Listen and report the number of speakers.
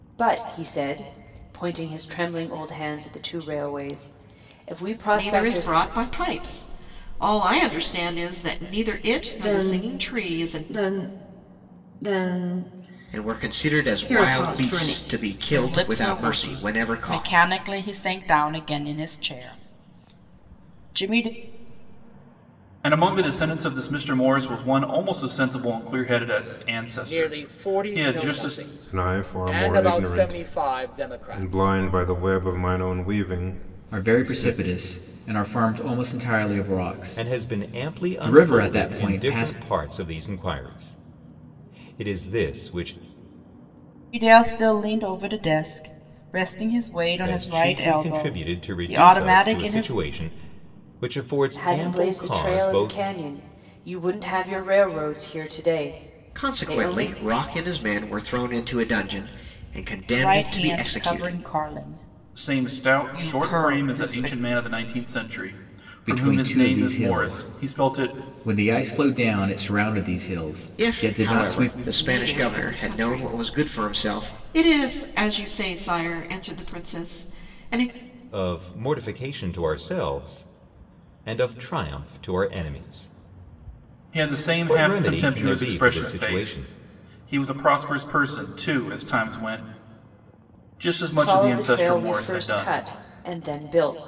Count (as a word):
ten